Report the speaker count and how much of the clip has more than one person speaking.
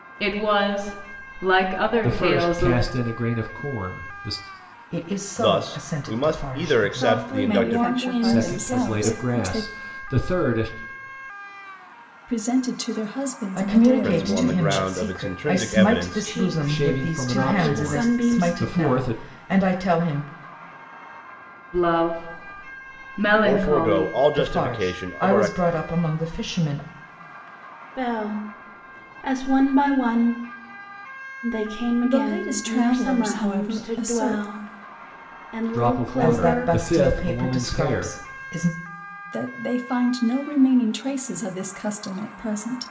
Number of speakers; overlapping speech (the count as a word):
six, about 41%